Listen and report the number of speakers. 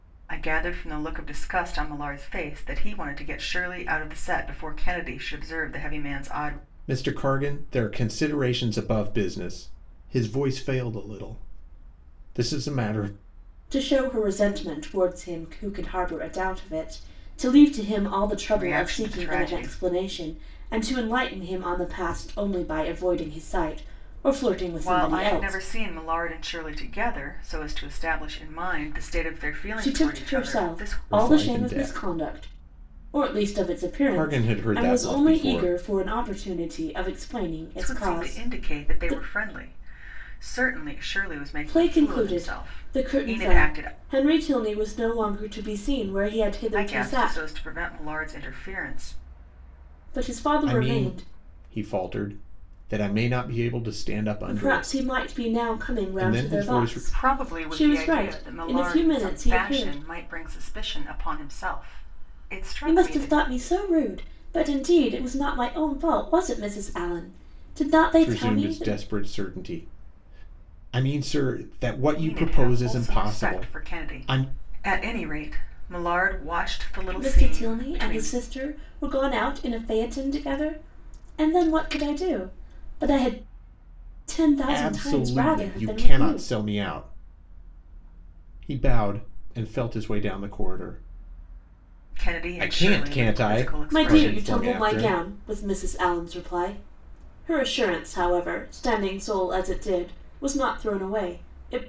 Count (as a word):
three